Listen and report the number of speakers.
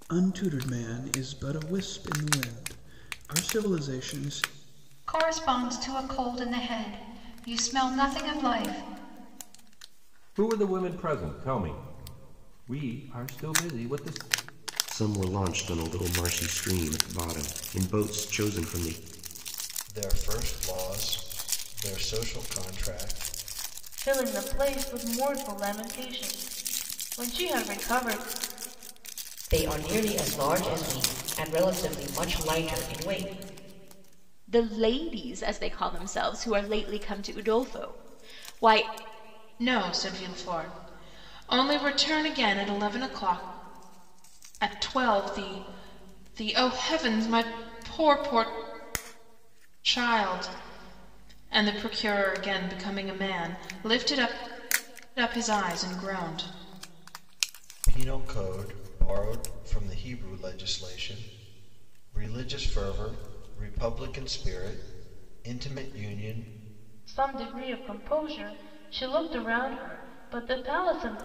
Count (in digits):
9